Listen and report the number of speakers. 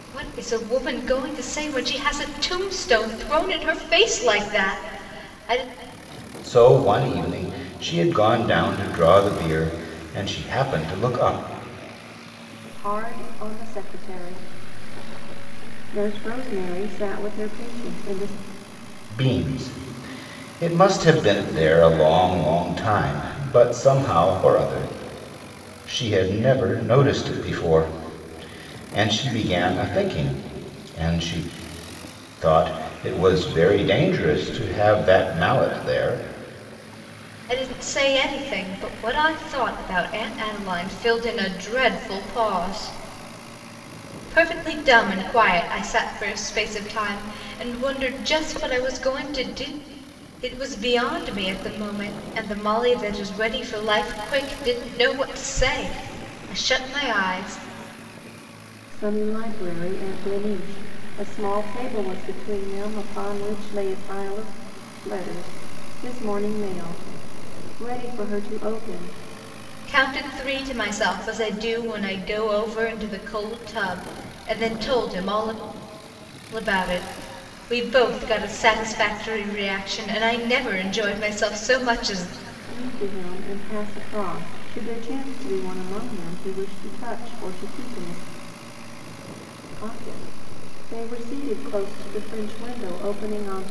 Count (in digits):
3